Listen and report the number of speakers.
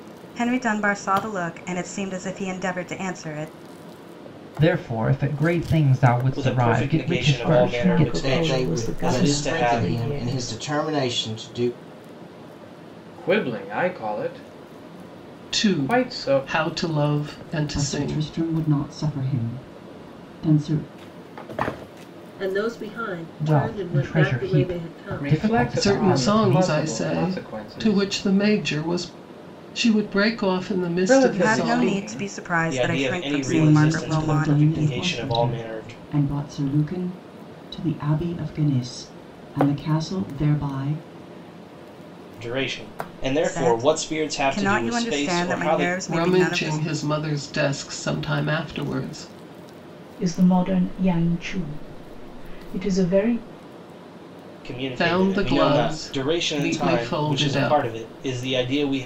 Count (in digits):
9